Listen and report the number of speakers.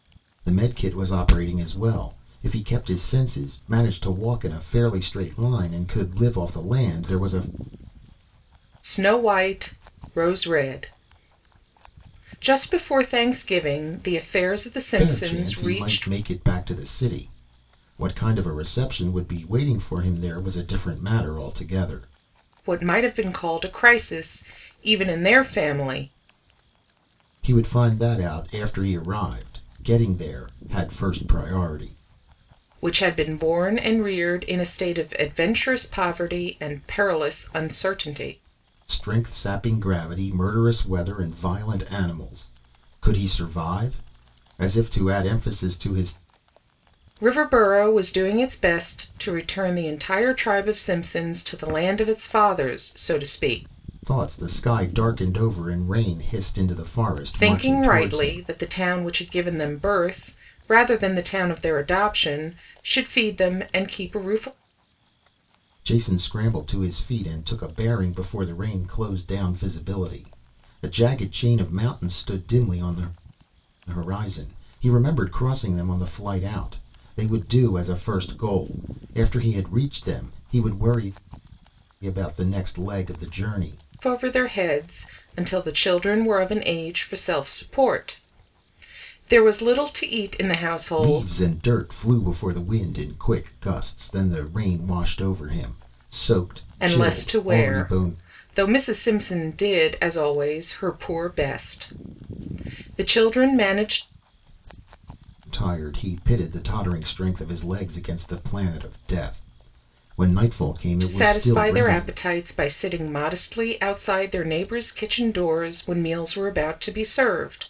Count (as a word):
two